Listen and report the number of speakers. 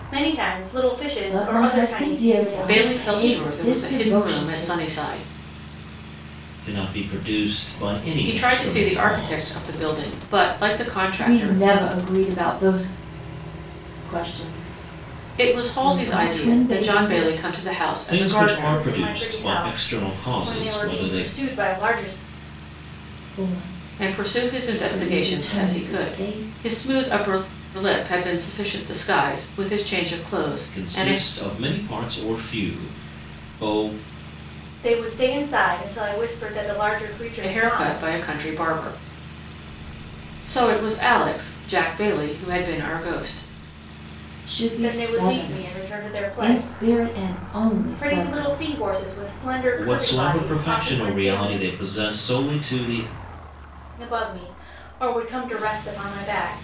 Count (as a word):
four